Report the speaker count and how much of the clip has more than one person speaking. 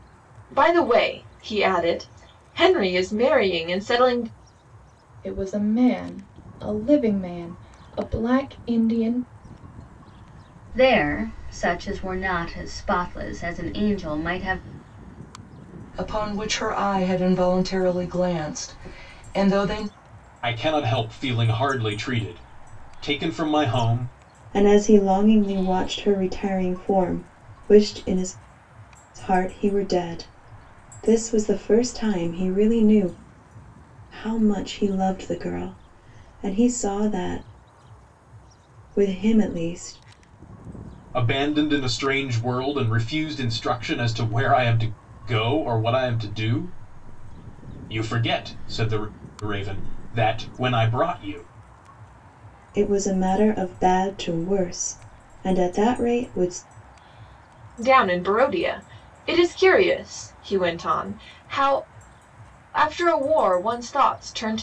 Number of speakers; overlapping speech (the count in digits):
6, no overlap